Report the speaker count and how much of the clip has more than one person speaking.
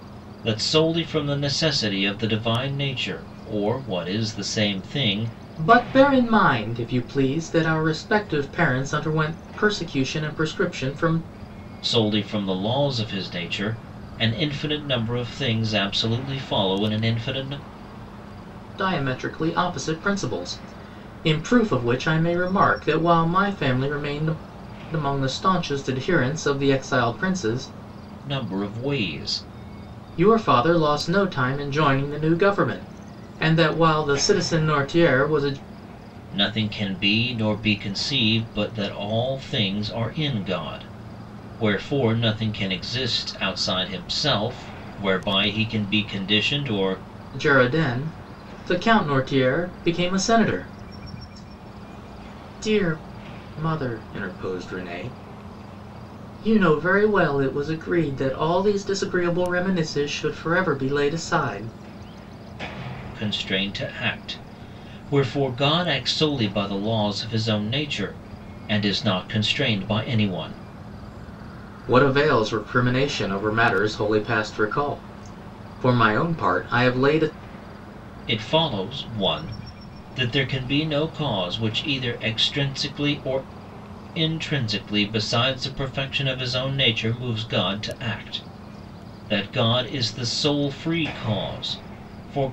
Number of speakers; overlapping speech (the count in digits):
2, no overlap